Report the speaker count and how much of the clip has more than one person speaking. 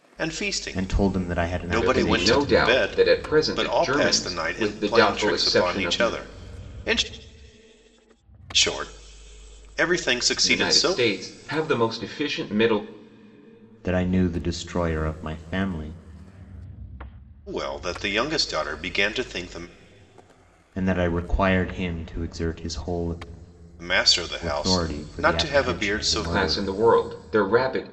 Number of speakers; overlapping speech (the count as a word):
three, about 30%